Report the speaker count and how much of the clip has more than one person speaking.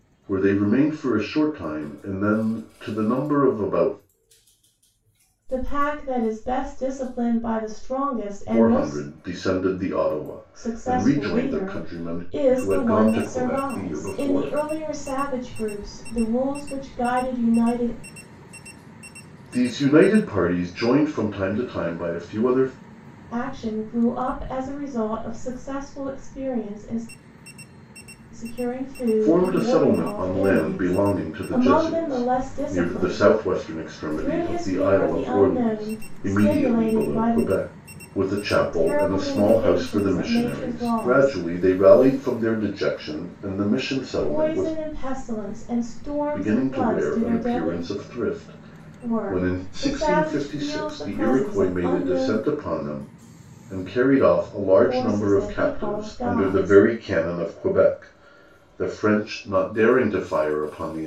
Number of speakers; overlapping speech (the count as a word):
two, about 37%